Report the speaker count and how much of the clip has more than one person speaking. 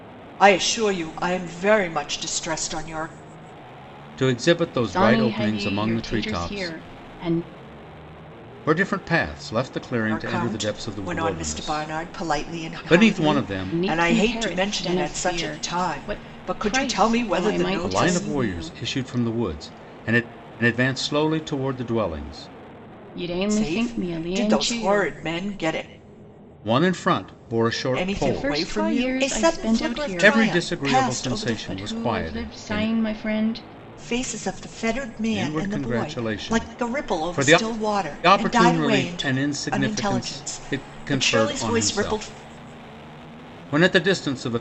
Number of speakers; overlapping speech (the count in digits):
3, about 51%